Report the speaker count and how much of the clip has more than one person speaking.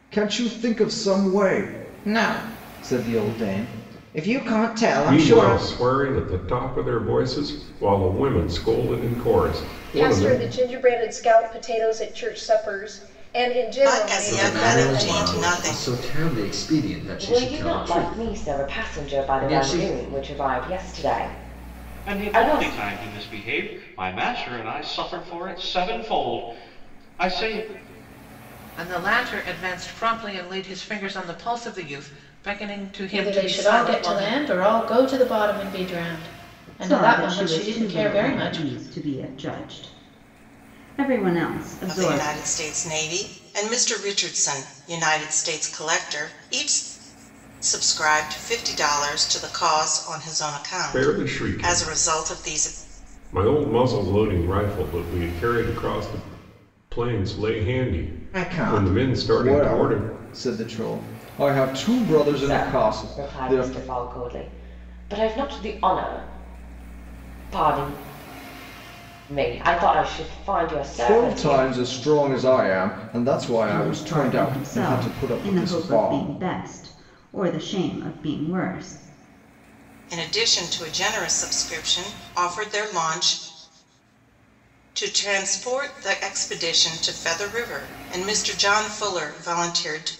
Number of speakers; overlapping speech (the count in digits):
10, about 21%